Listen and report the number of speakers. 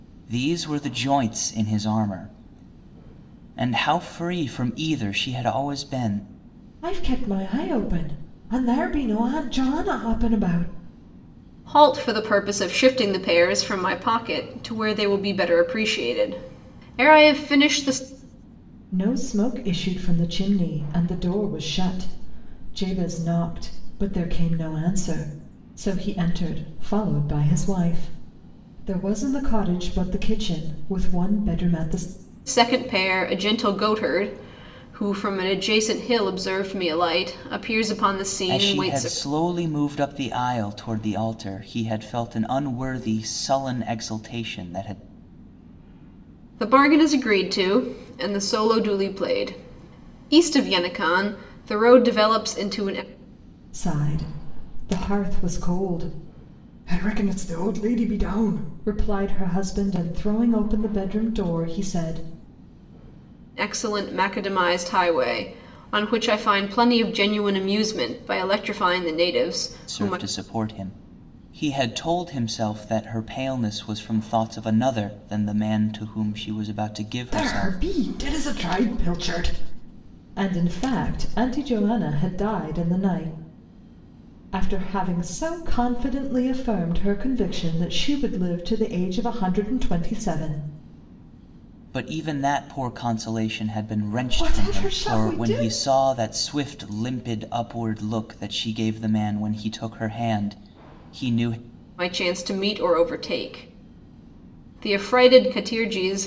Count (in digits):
3